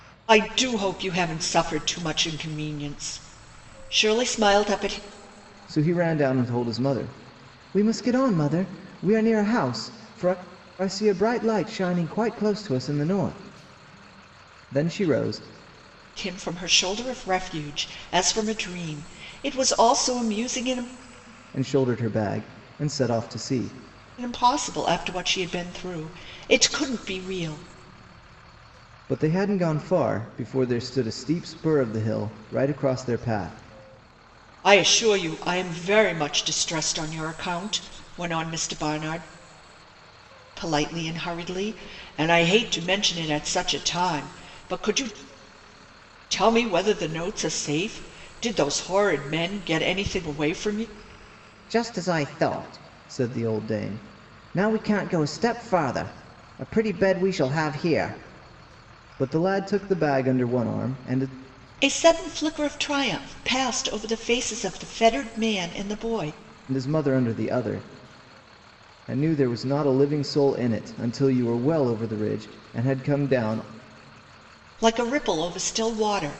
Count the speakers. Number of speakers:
two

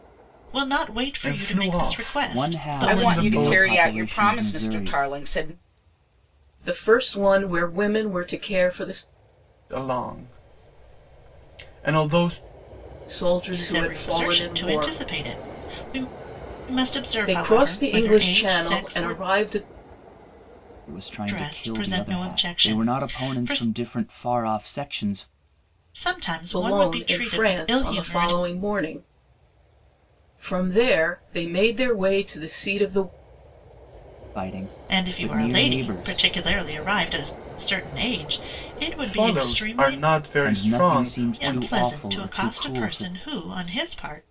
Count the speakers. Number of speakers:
five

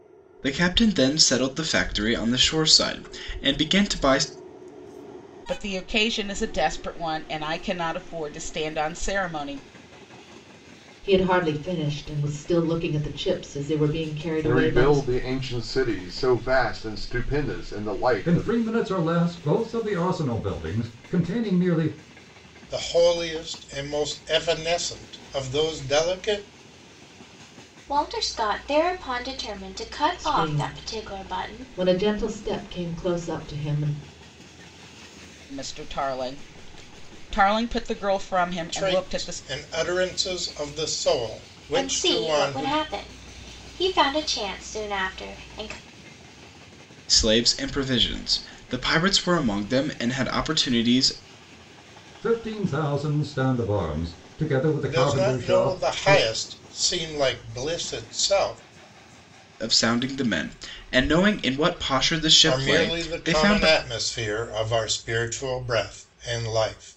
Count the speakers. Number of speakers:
seven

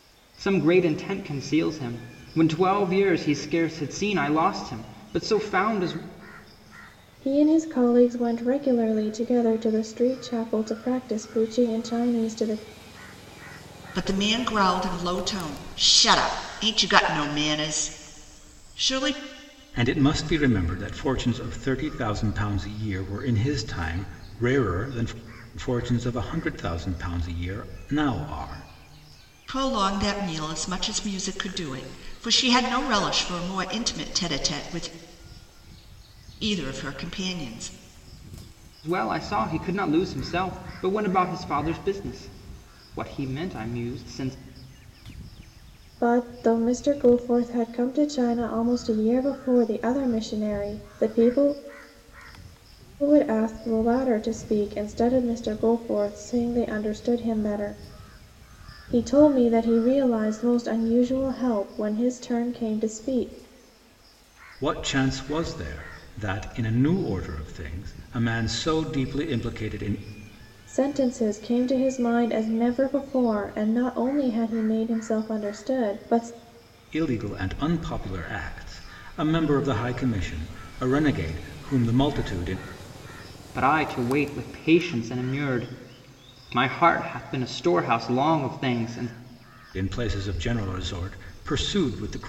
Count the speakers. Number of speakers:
four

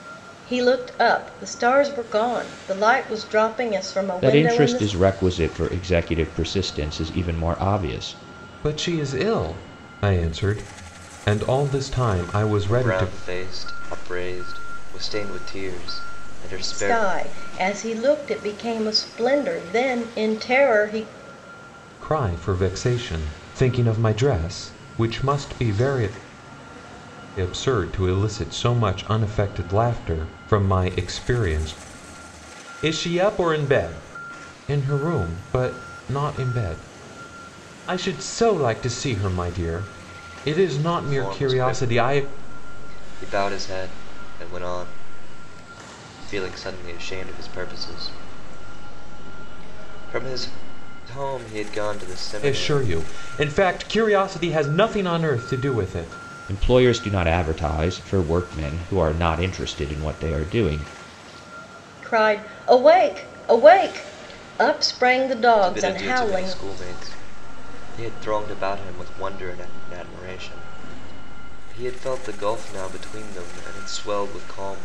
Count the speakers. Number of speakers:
four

